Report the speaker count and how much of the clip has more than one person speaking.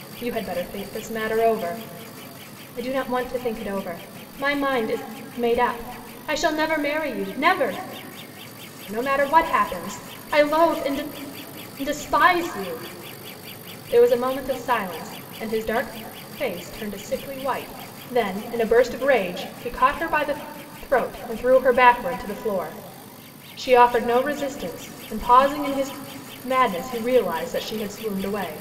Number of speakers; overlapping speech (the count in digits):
1, no overlap